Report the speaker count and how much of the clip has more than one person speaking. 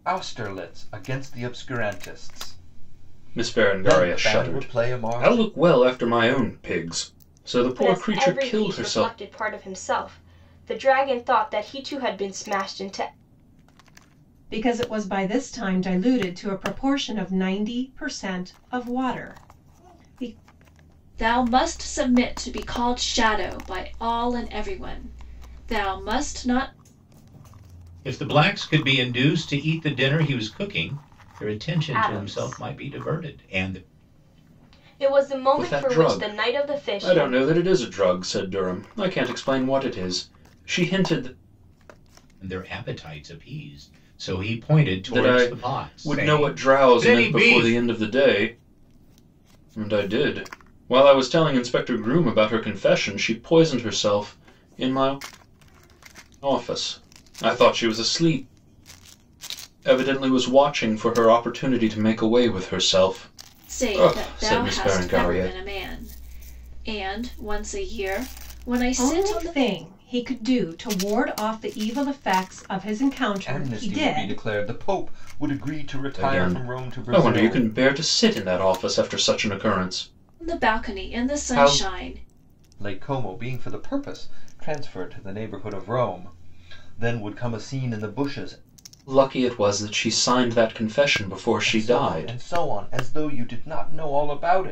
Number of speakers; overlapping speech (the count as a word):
six, about 18%